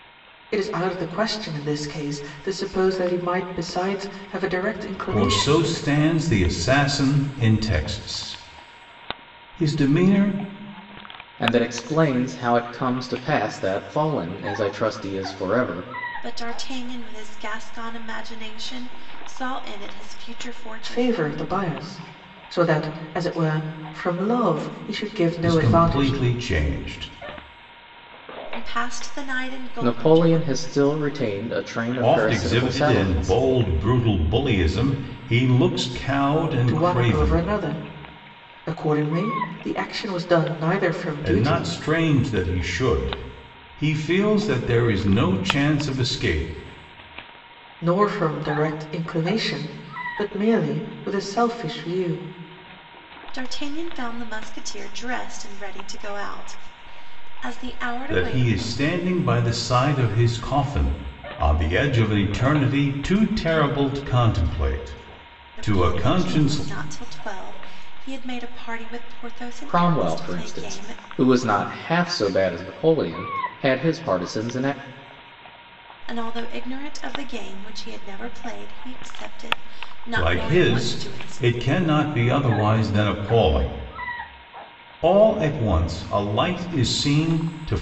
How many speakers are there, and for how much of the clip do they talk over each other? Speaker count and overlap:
4, about 11%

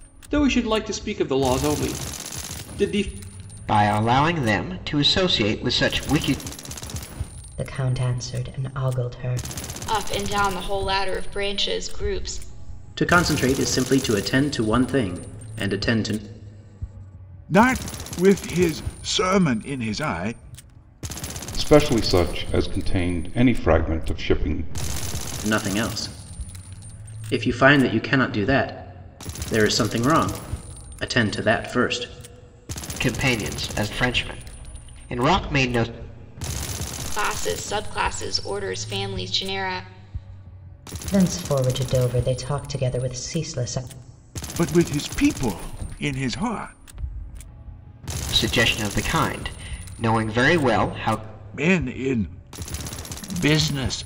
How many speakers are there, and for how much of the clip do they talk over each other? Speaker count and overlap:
7, no overlap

